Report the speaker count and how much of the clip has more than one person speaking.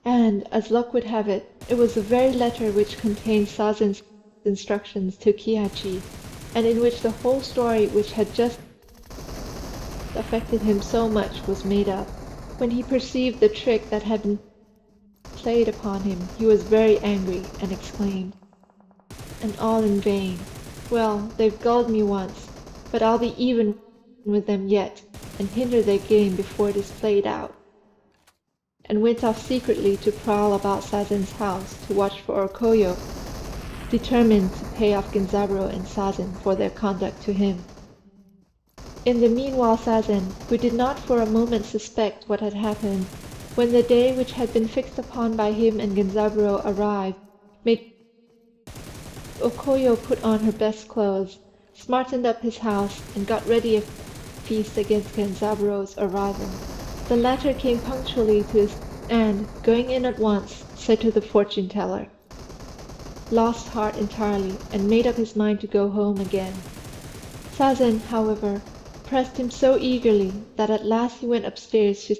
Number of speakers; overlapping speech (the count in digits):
1, no overlap